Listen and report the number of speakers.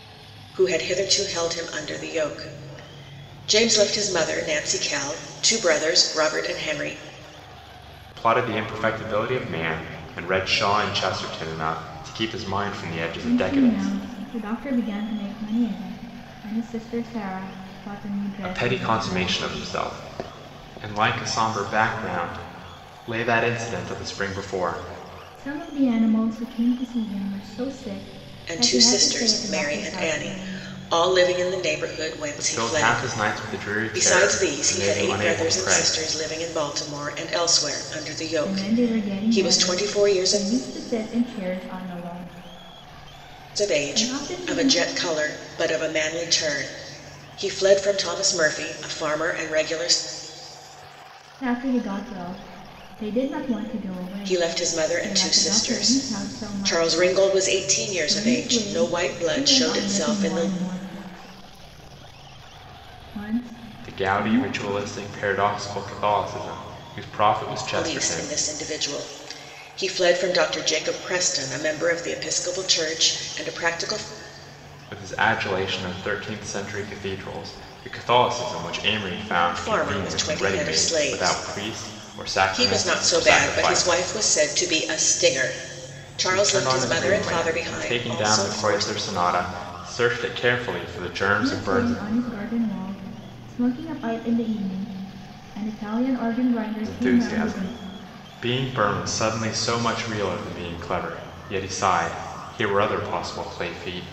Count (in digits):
3